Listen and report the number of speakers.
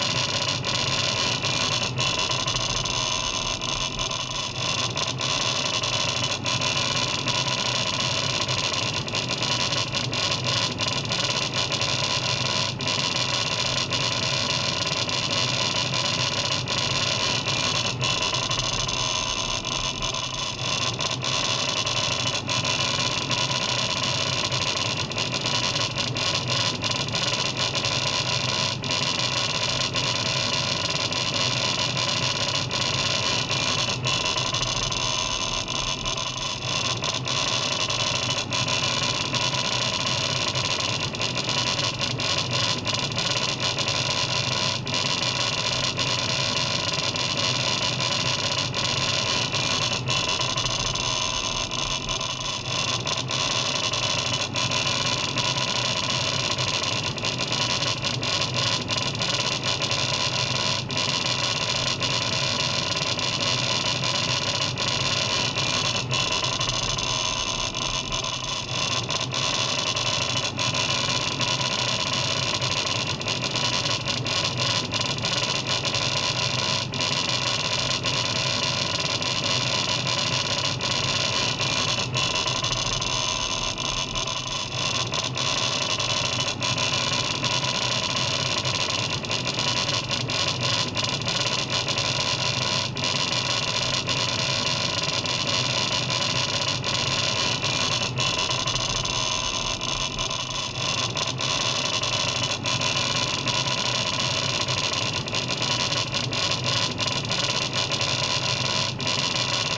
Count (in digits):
0